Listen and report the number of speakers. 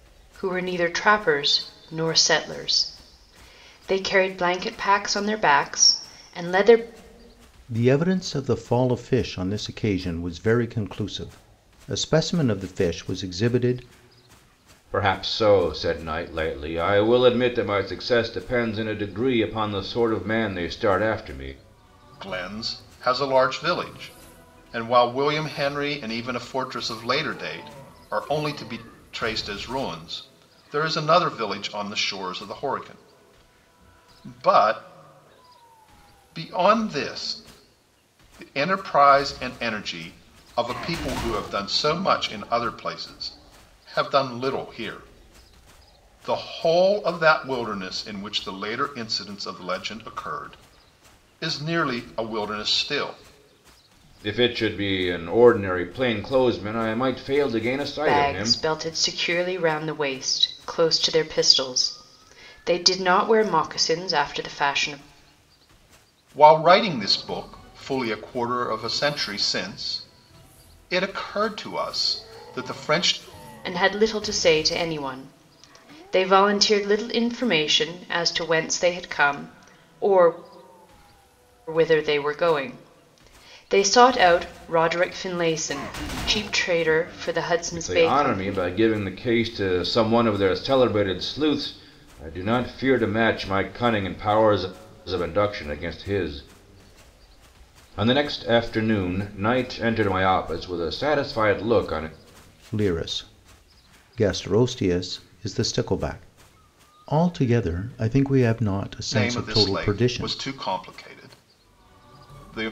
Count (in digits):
4